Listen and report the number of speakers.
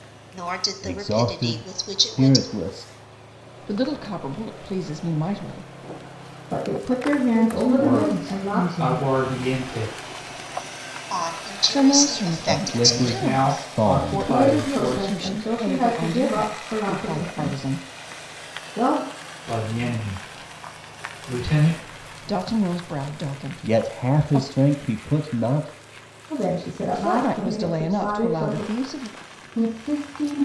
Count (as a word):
six